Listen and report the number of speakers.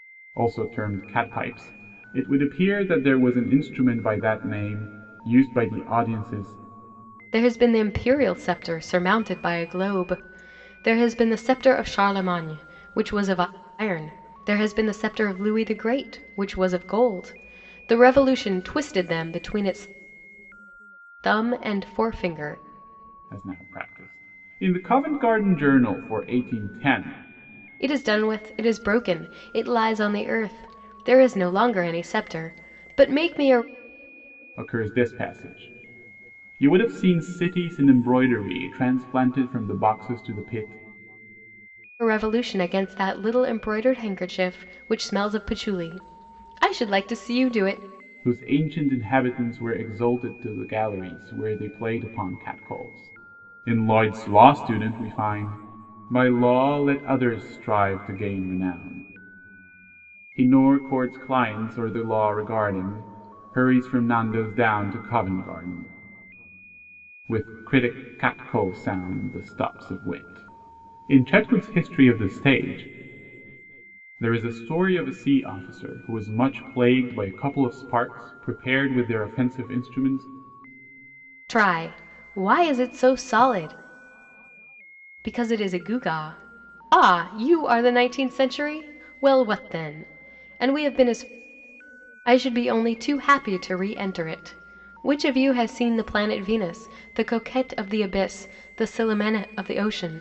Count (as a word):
two